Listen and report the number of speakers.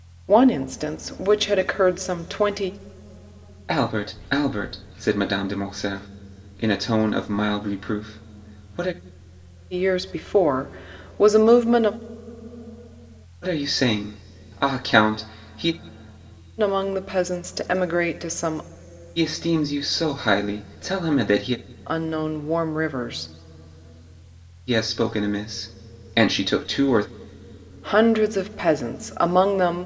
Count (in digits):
2